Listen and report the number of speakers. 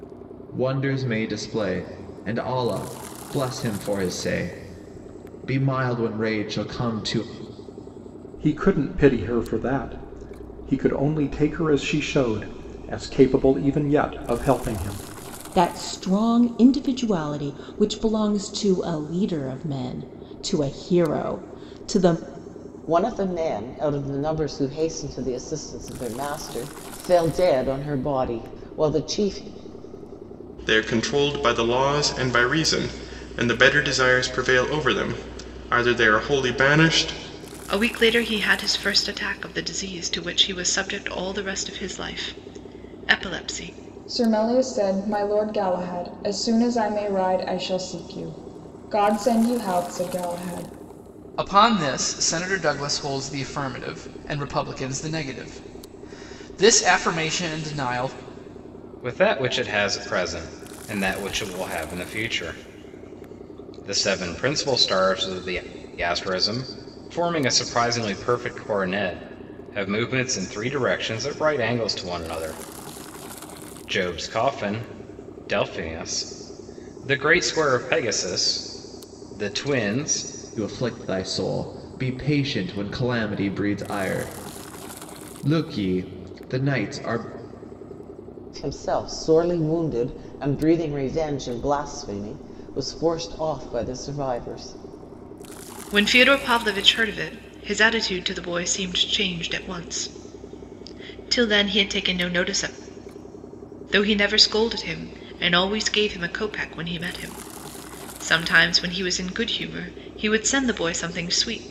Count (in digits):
9